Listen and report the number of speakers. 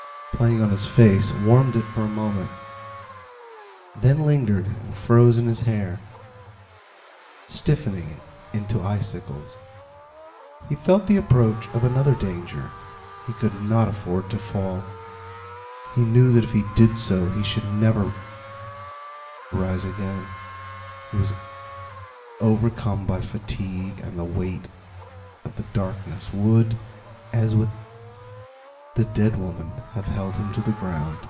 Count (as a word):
one